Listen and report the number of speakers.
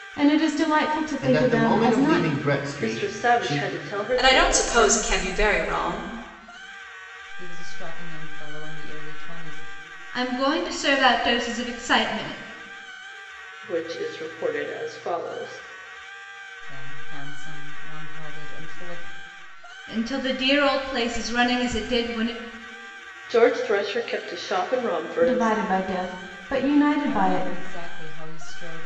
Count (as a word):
six